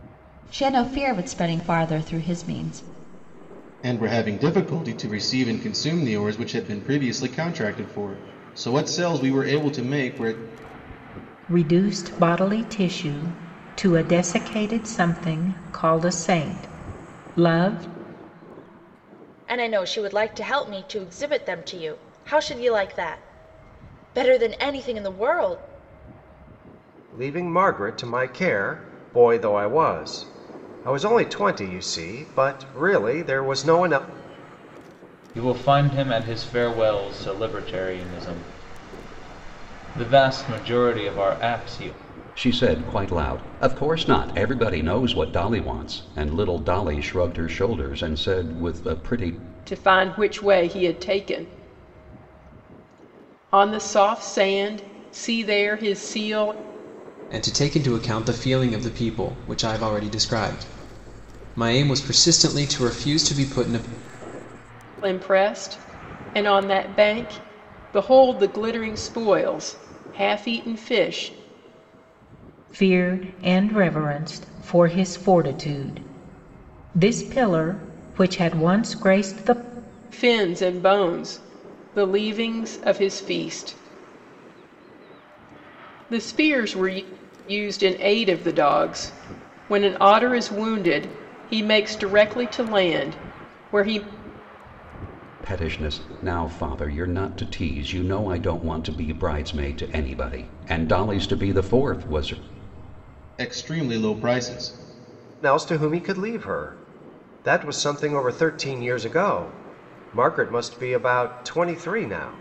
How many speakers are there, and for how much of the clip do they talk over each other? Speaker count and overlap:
9, no overlap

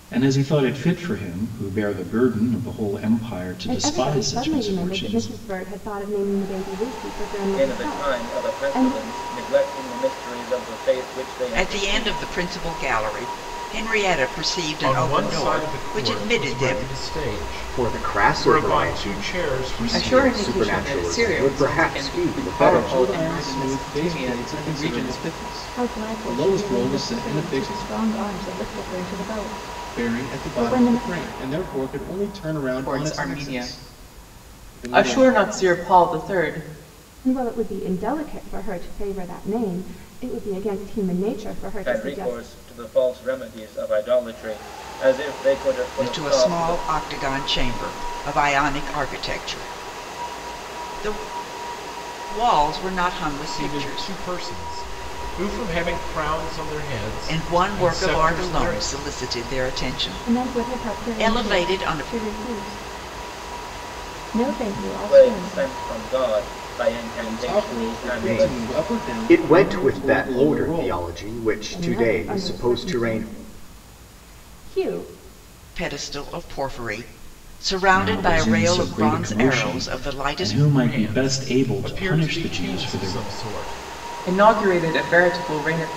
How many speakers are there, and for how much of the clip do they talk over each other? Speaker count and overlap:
9, about 42%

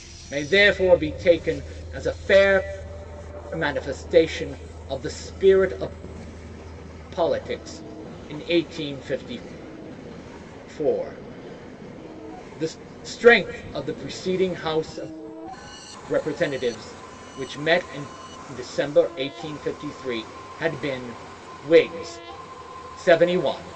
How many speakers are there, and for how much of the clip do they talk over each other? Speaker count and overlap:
1, no overlap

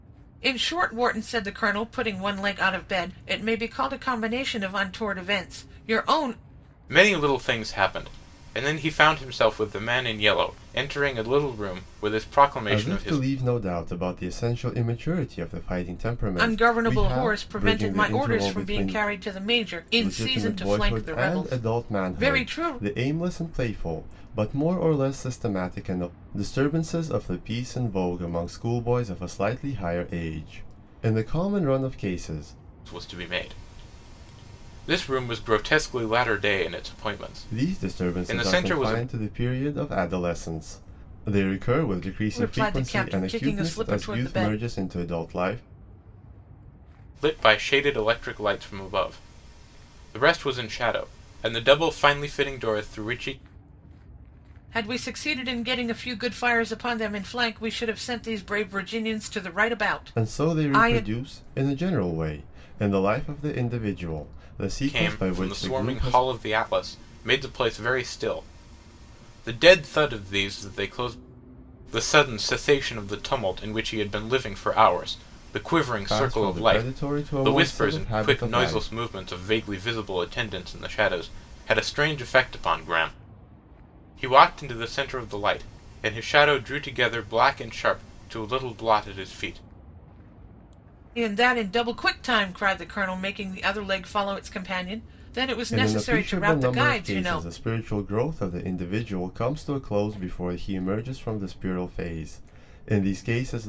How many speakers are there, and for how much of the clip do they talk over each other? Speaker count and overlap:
3, about 17%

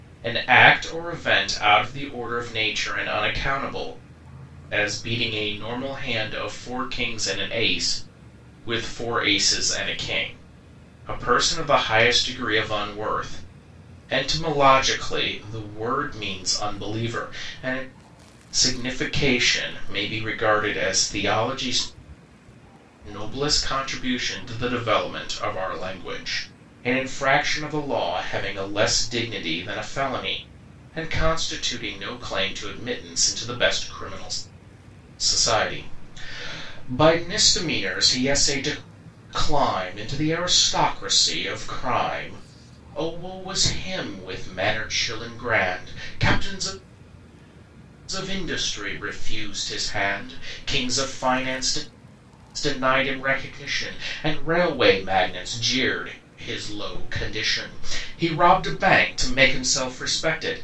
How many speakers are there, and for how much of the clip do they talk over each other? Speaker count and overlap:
1, no overlap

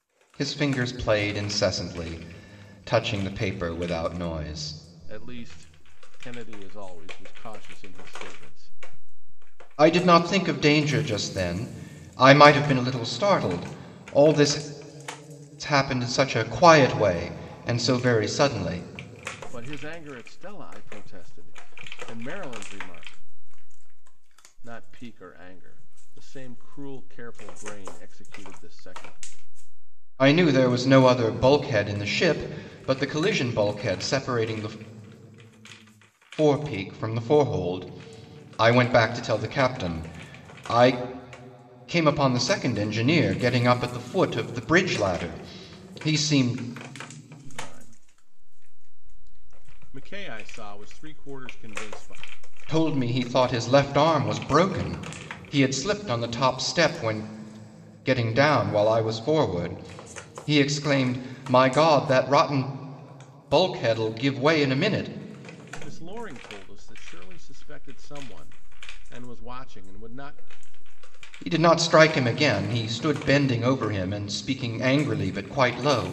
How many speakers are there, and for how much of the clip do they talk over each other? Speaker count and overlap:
2, no overlap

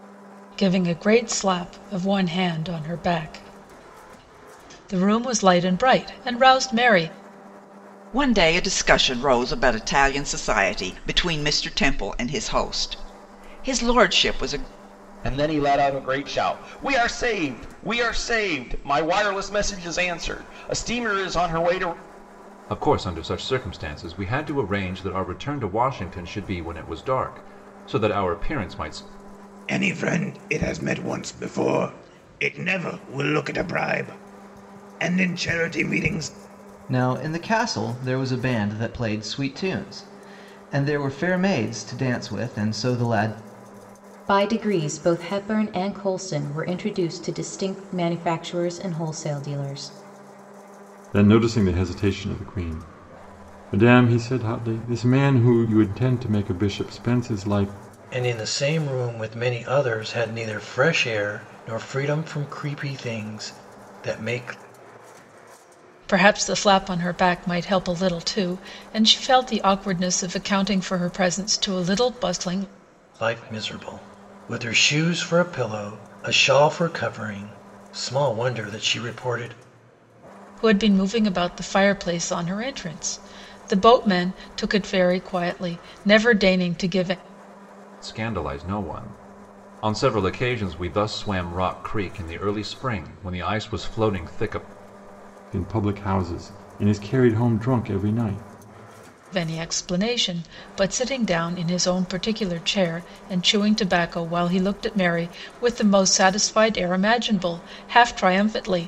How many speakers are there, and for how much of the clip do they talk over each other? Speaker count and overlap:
9, no overlap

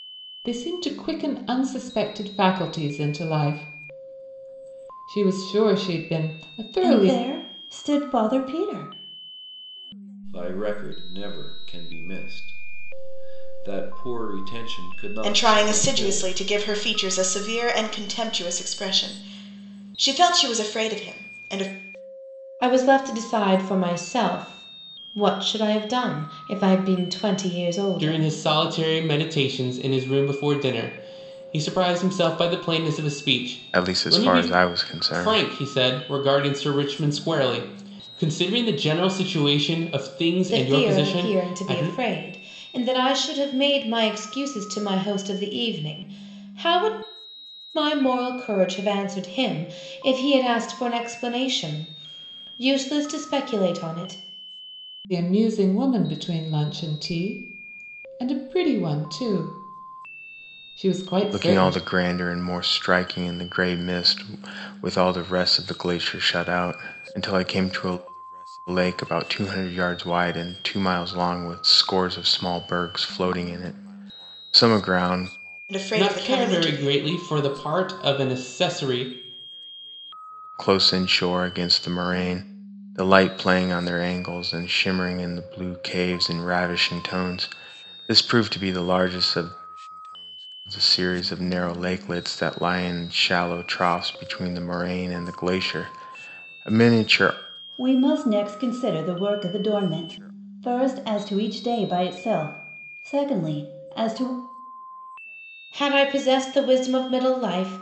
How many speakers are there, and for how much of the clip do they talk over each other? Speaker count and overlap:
7, about 6%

